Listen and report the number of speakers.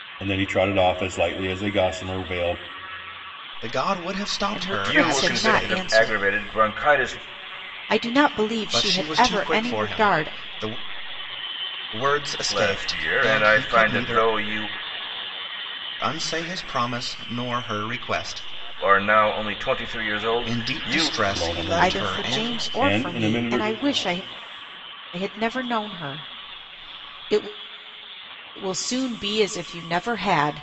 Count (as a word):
four